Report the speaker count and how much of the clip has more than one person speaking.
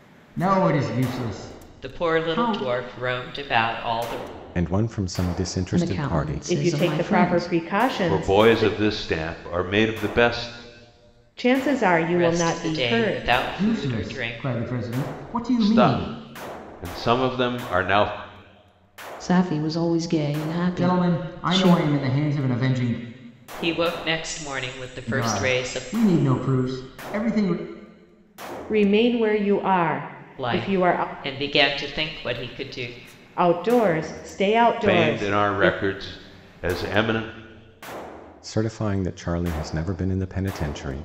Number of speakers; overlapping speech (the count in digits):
6, about 24%